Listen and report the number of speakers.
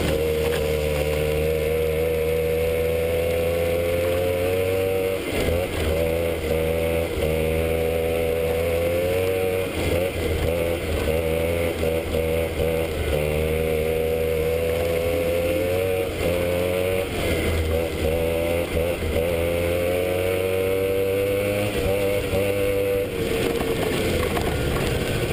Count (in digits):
0